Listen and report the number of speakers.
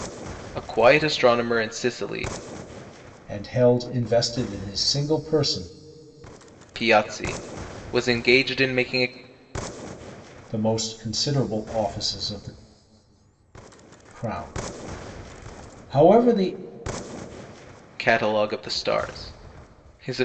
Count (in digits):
2